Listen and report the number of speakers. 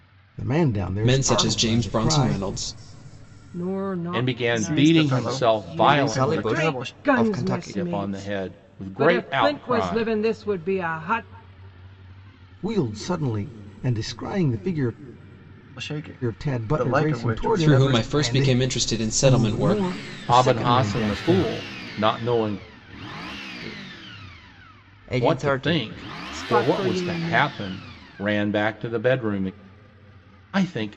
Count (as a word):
six